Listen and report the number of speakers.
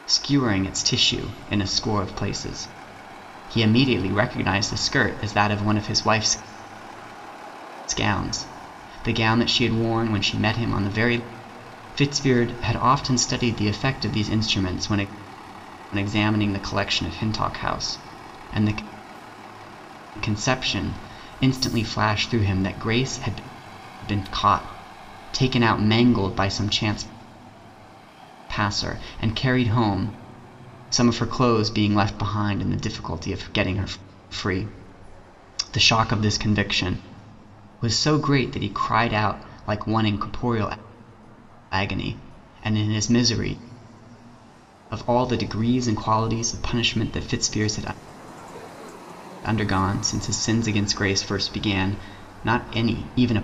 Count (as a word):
one